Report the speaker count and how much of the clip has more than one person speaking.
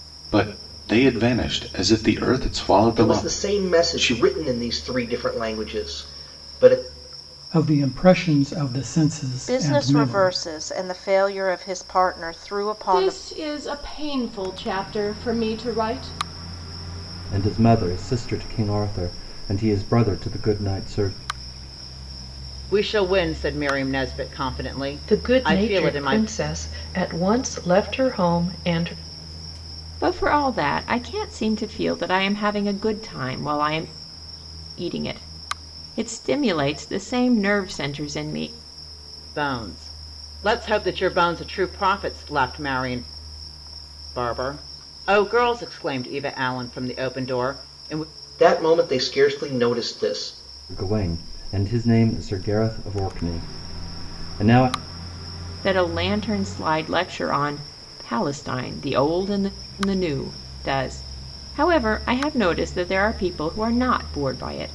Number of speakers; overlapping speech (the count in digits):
9, about 6%